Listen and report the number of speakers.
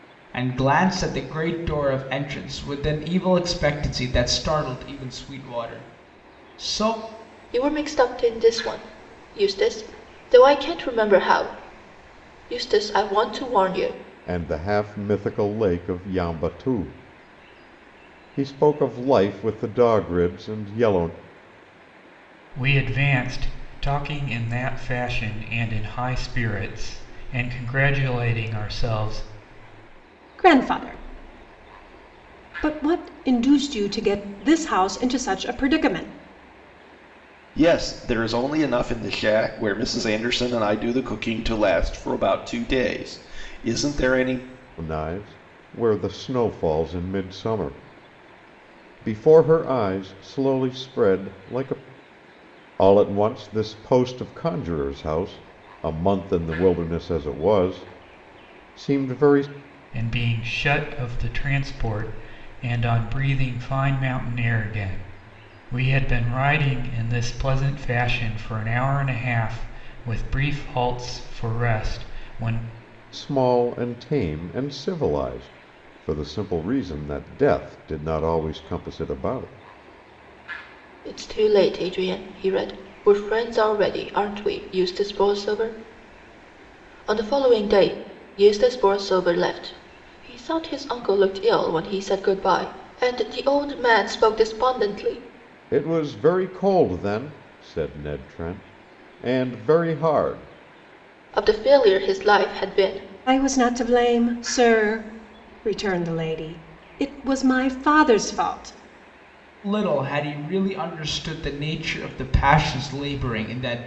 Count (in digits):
6